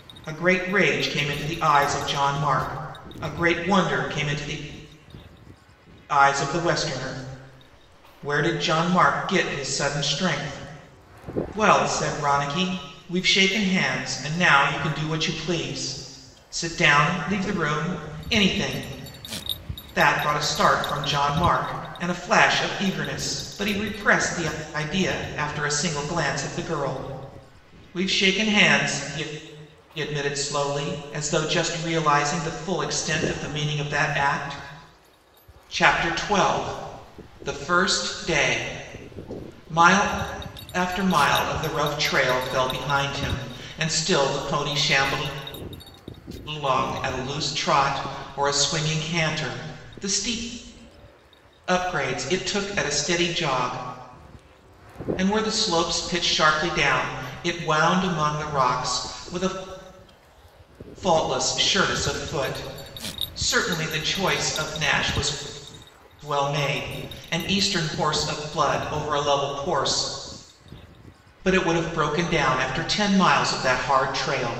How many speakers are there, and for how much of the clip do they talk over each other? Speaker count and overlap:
1, no overlap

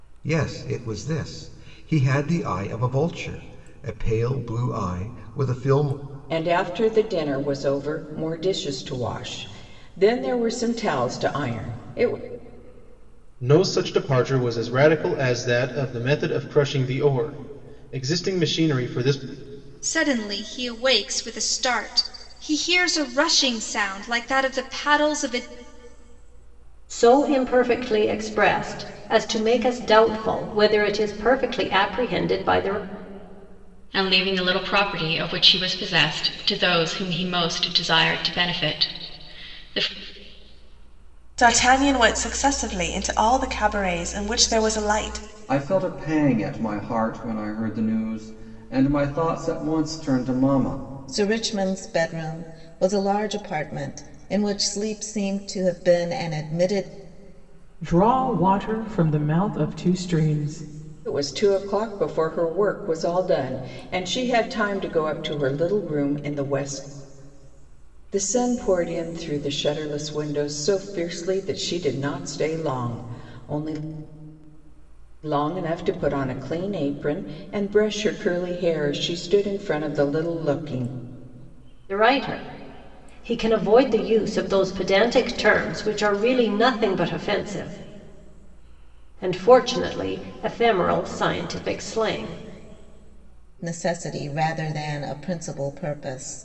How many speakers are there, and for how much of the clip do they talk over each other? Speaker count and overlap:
10, no overlap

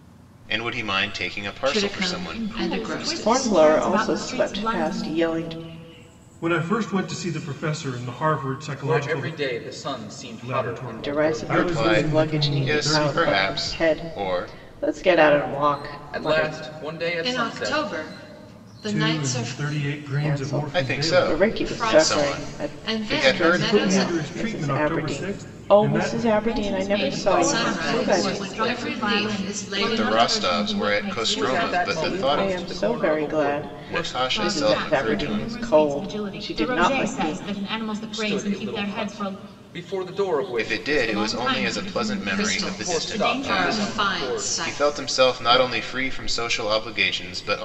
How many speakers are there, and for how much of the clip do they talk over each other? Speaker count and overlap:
6, about 70%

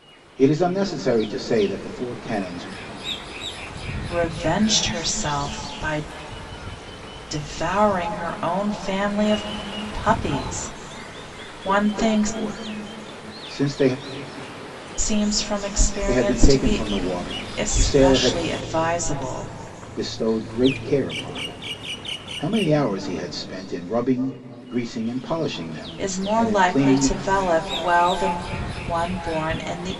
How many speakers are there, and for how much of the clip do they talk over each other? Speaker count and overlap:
2, about 12%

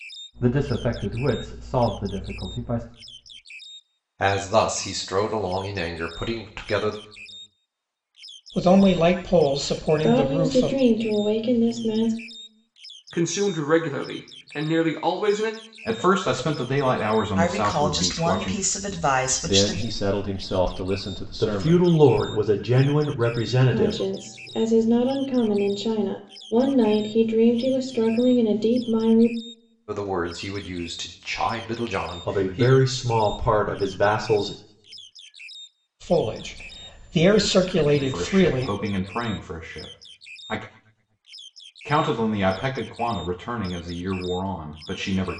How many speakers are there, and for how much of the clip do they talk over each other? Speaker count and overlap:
9, about 10%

